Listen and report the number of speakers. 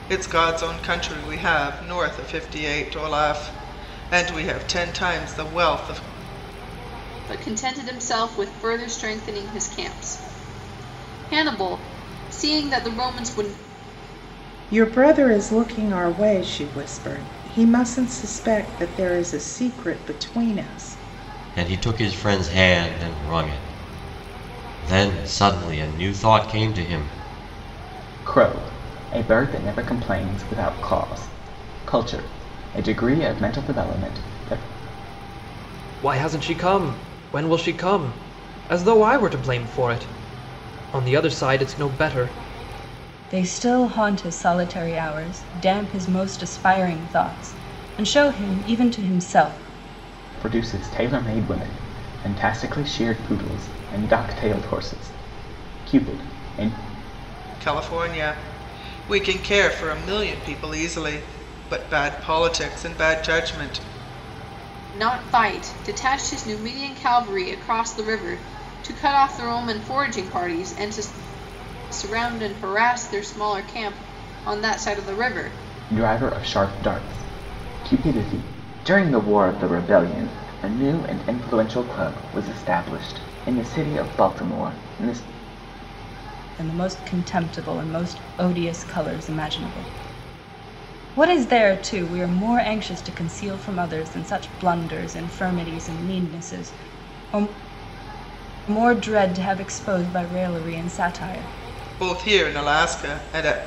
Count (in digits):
7